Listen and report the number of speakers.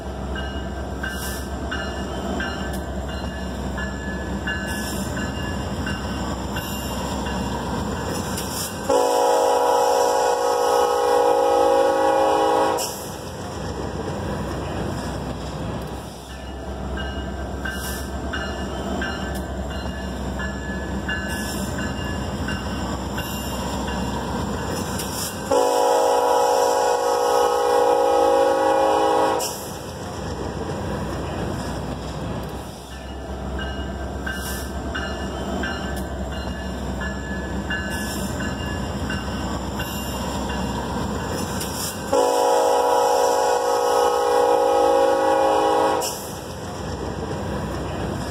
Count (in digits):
0